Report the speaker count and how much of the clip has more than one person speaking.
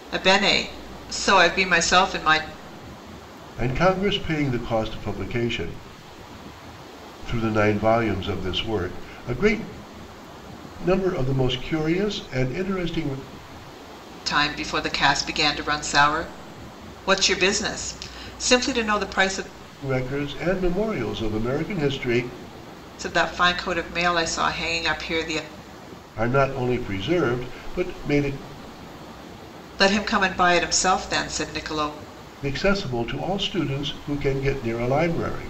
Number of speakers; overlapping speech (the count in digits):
2, no overlap